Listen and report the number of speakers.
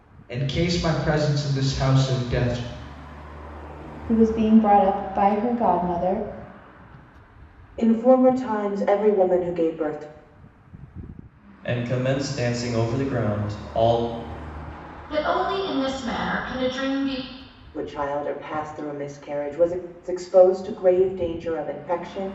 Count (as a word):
five